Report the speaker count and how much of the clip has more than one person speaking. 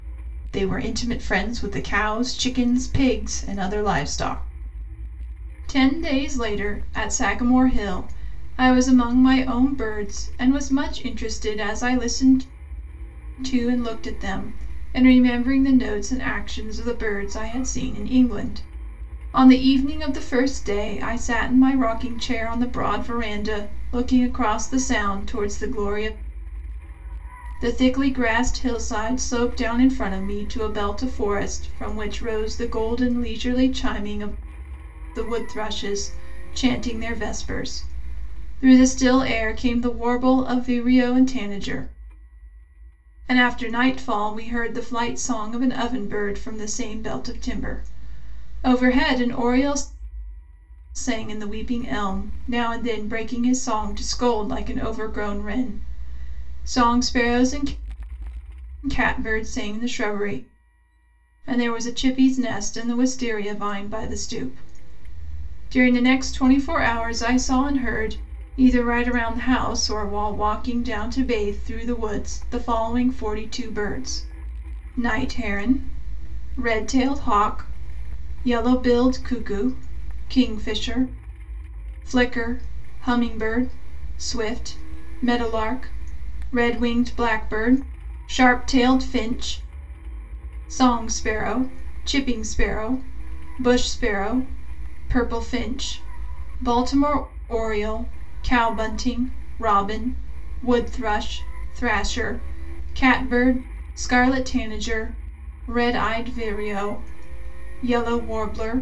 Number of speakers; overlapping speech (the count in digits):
1, no overlap